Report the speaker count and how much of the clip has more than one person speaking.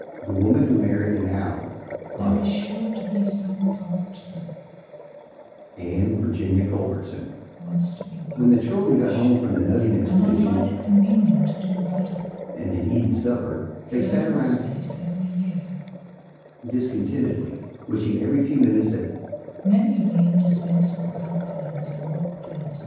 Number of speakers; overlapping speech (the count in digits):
2, about 12%